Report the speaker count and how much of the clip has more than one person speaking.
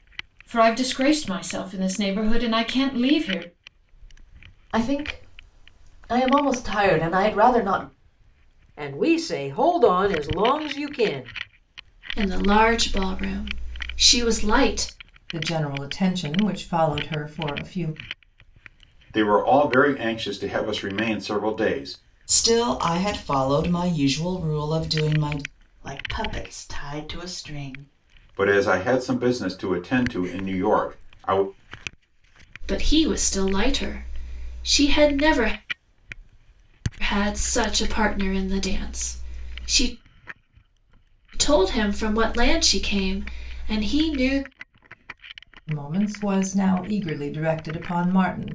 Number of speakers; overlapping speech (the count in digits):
8, no overlap